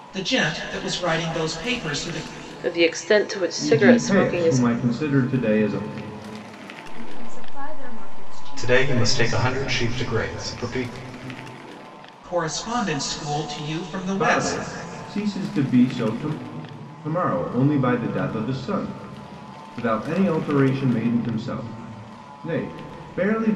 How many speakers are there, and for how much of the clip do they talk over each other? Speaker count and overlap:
5, about 10%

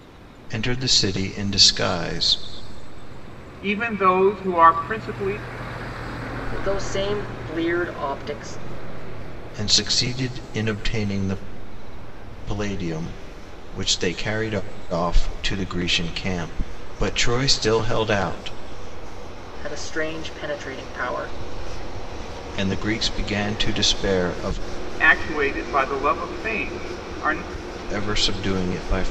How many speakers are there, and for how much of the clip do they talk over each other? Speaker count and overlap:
3, no overlap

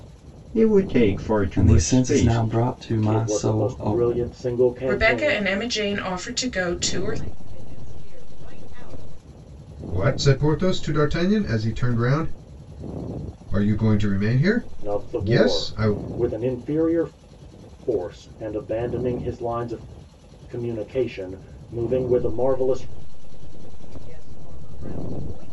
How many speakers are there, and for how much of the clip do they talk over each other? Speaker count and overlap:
6, about 19%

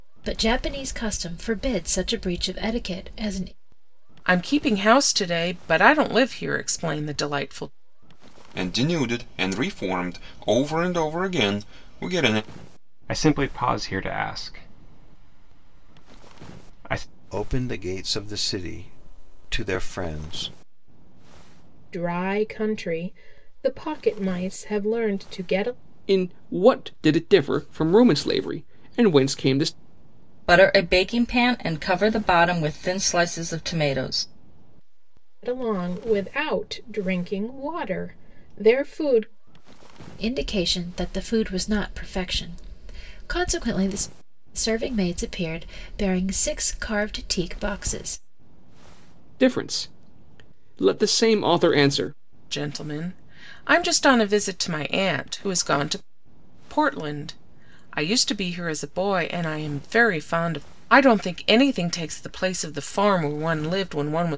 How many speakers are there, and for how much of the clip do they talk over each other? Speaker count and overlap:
8, no overlap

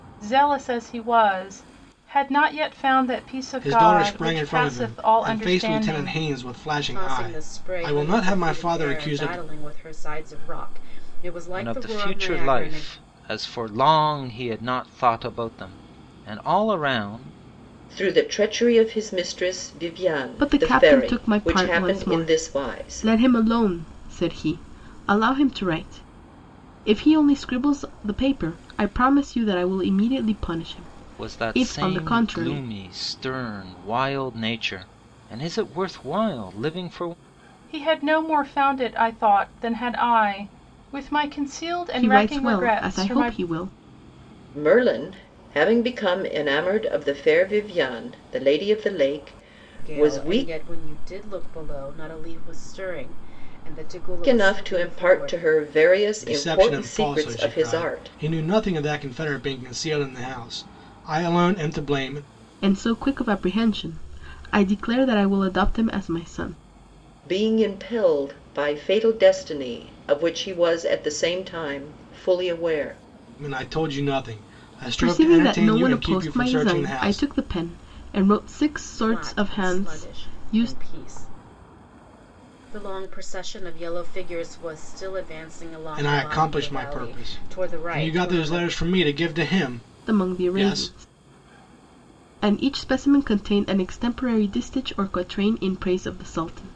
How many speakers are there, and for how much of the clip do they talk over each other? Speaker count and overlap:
6, about 25%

